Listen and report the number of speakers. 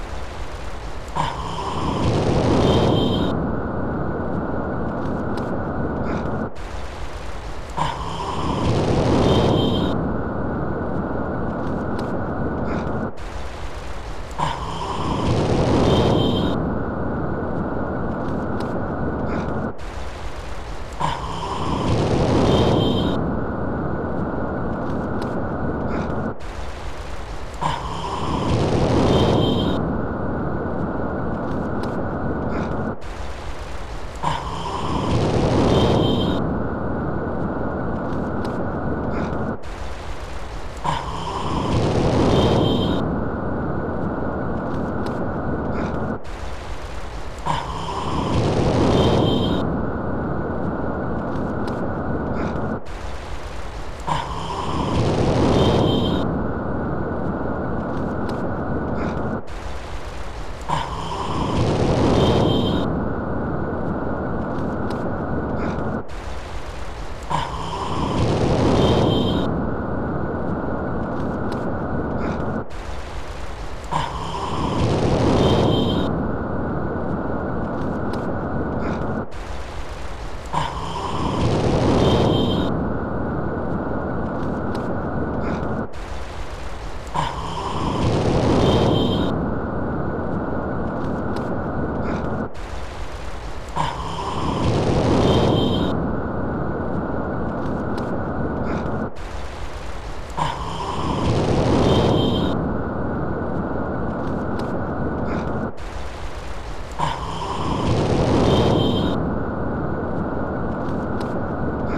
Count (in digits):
0